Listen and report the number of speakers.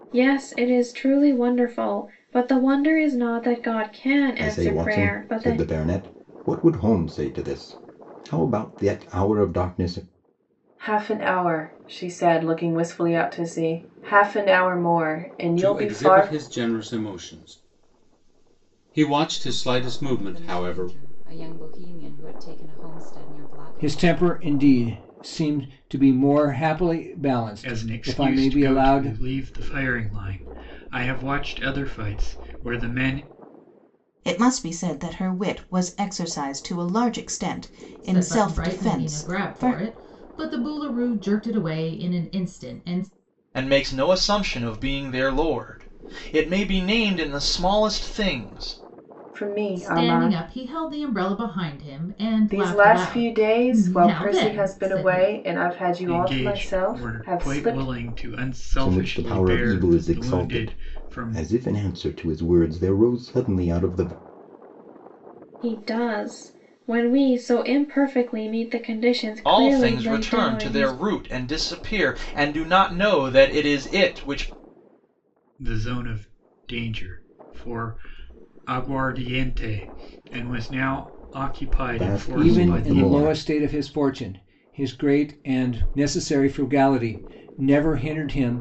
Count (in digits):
10